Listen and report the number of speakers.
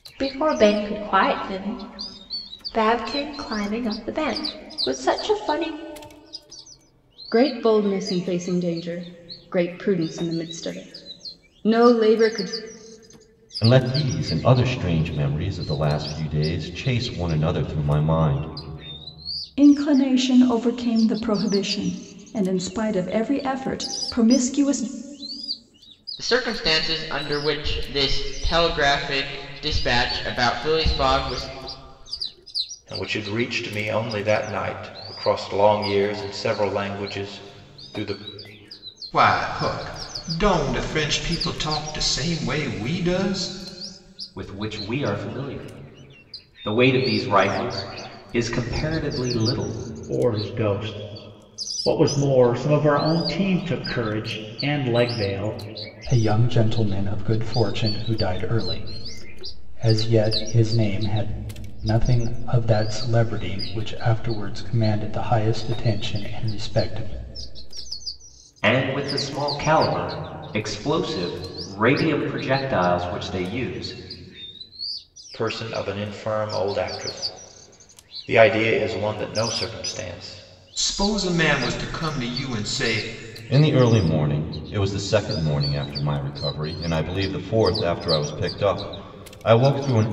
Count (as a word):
ten